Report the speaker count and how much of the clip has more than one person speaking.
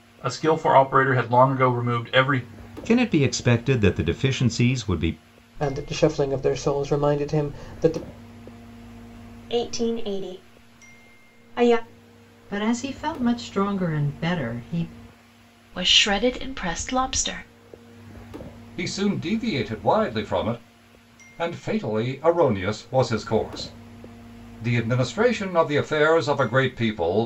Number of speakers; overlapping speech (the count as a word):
seven, no overlap